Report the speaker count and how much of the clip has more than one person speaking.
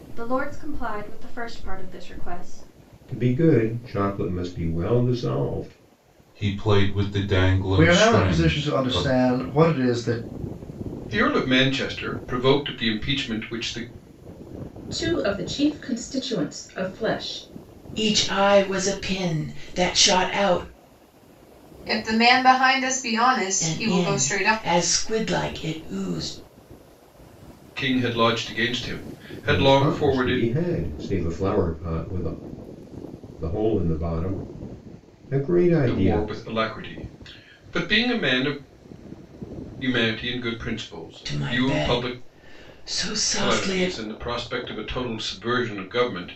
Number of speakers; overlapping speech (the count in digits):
8, about 12%